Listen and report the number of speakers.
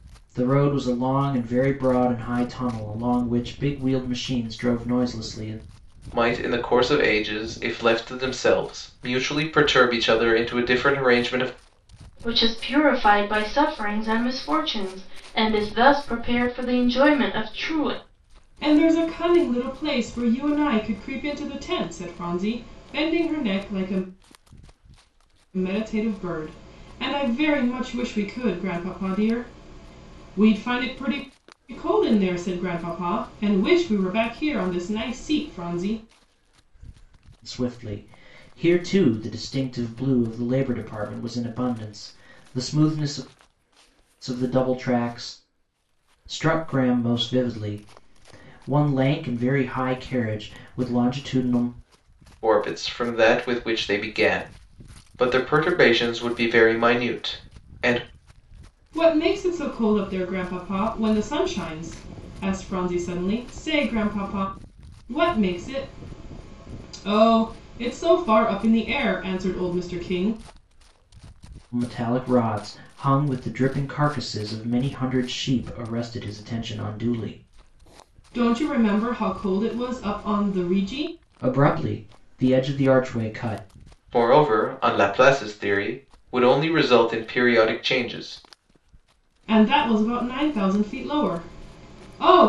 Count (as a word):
four